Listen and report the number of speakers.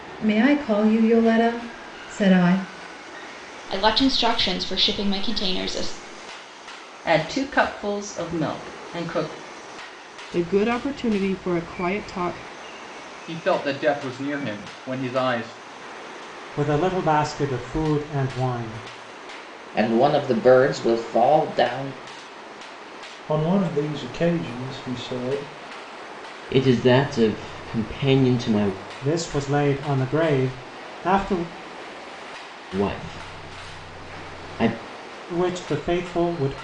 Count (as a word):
nine